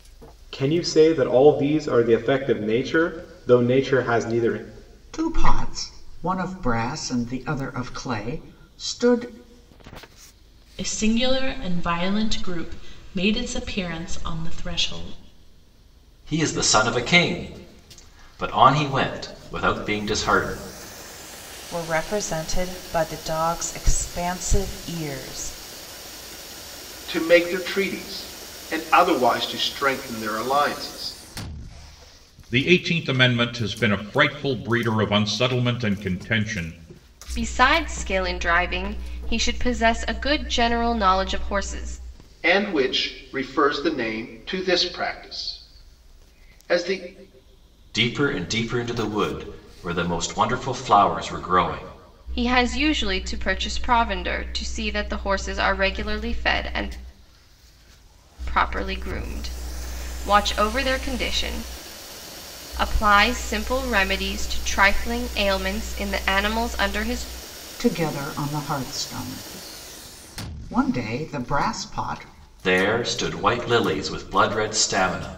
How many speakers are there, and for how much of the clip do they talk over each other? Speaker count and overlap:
eight, no overlap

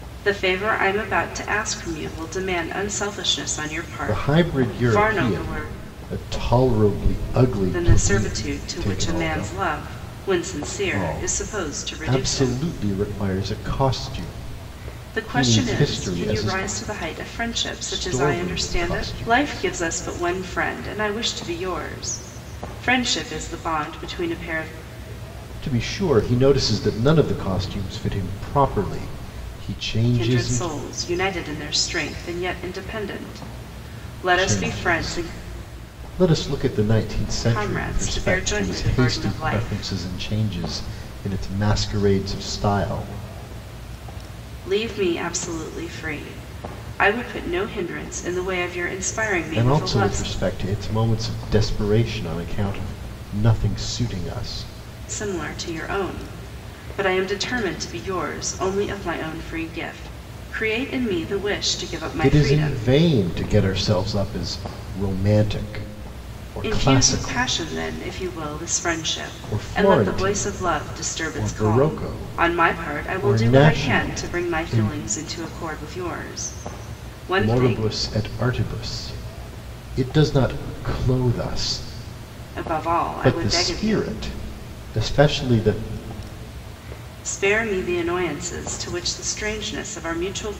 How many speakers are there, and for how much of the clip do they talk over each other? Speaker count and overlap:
two, about 24%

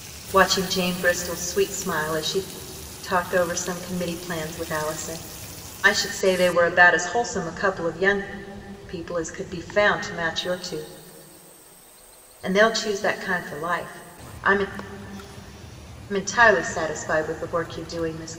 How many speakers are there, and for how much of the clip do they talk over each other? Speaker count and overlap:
one, no overlap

